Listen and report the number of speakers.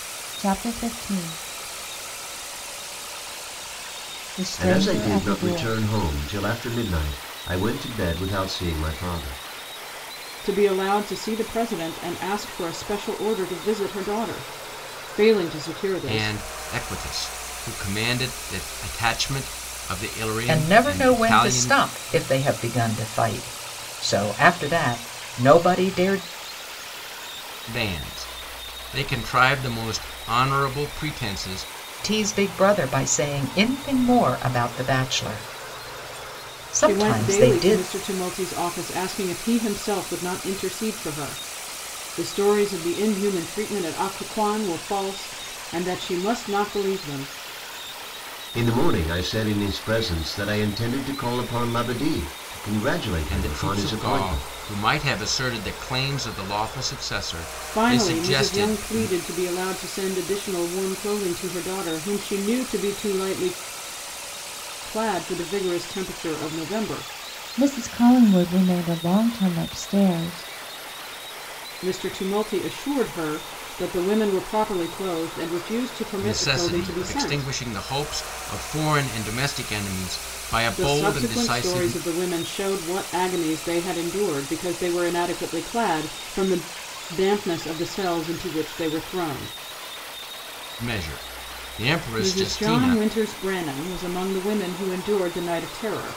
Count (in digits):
5